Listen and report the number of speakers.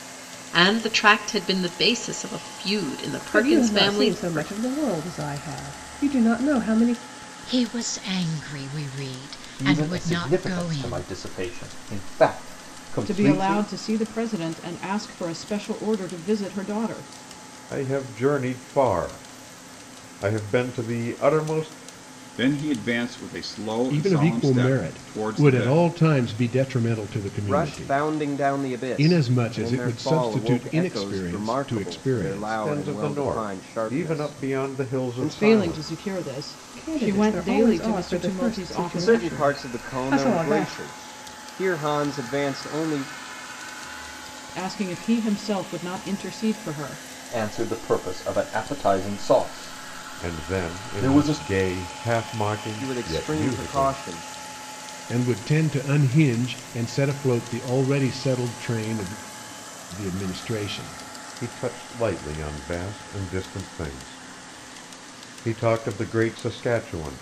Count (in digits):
9